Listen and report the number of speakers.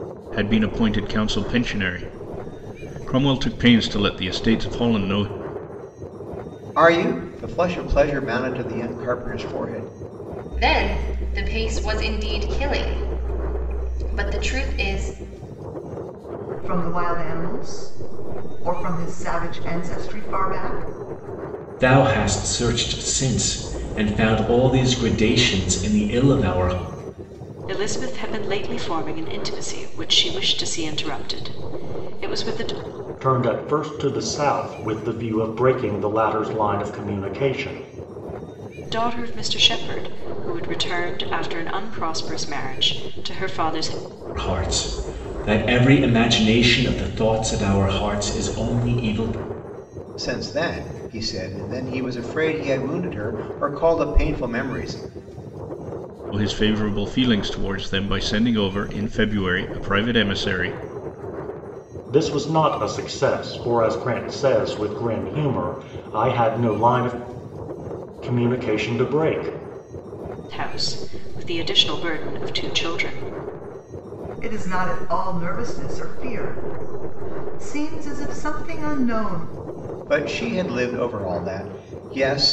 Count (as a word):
seven